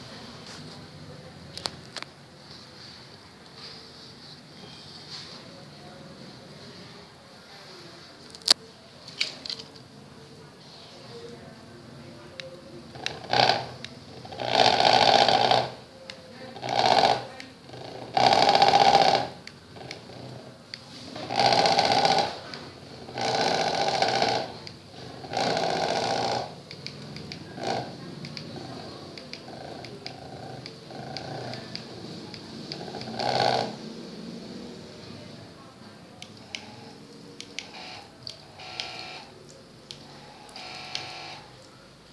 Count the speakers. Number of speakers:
0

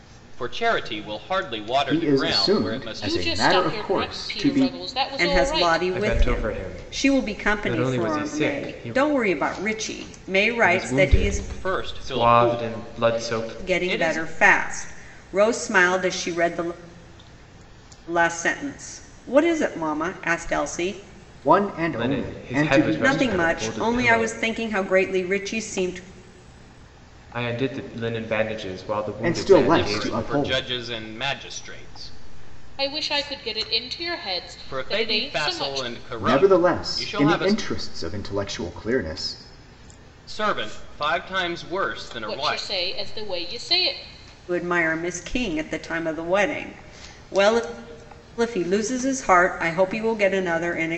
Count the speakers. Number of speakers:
5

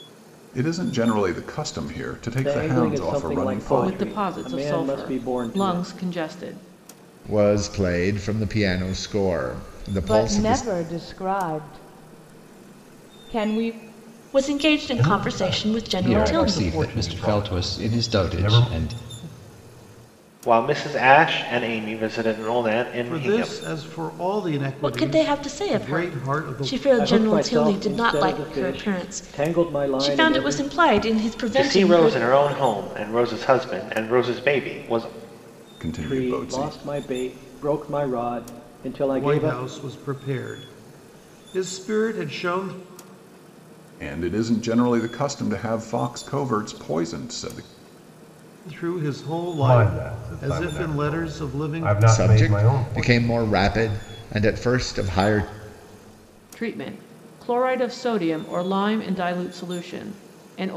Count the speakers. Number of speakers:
10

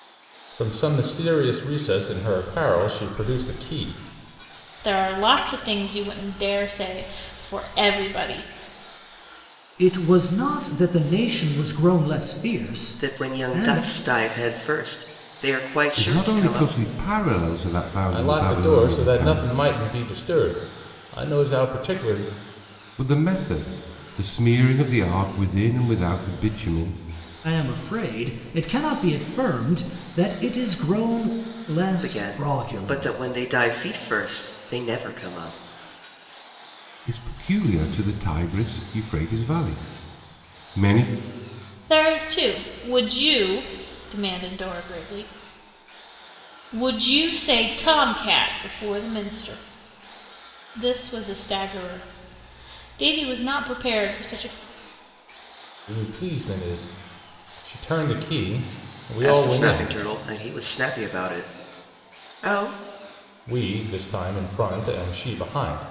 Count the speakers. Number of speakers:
5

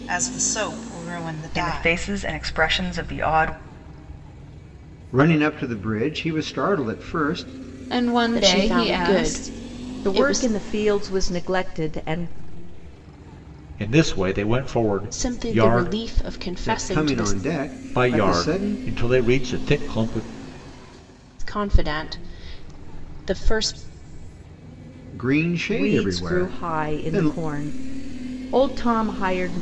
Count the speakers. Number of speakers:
7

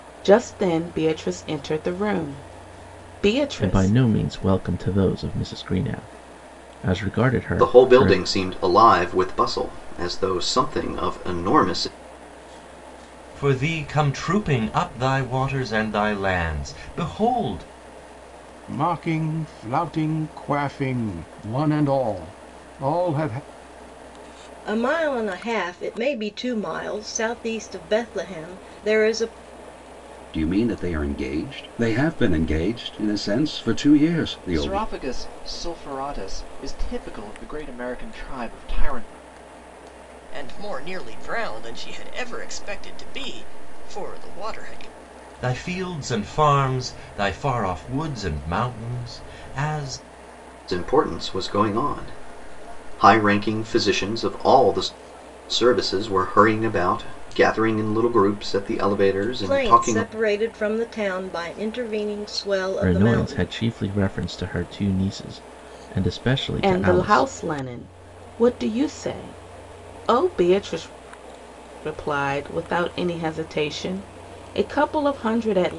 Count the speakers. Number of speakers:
9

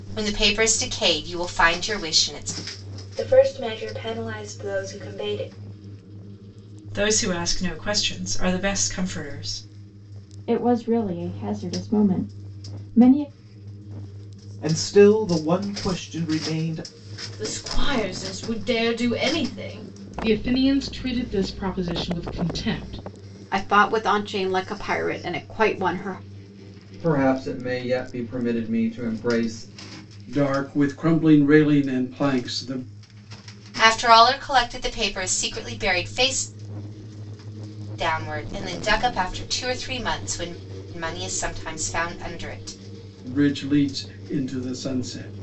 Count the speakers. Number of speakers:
10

